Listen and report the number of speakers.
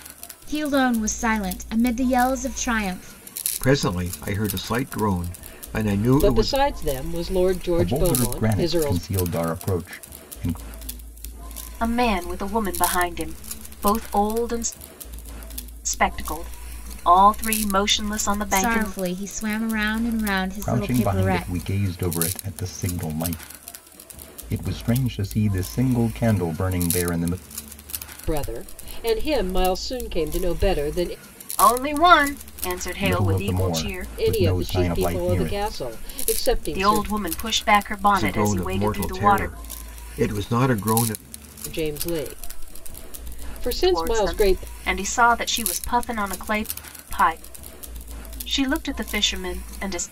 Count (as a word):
five